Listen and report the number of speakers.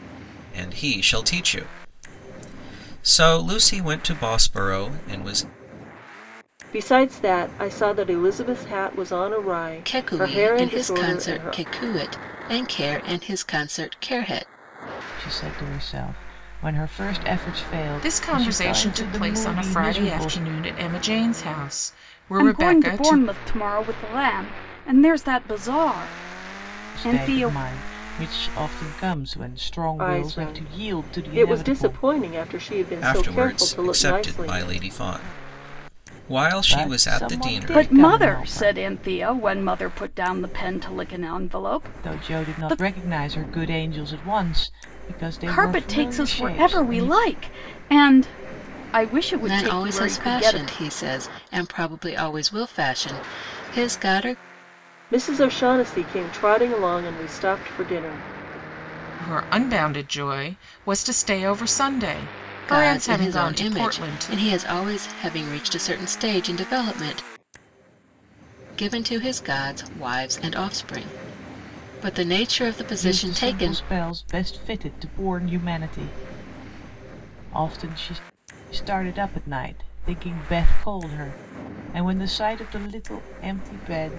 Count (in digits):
6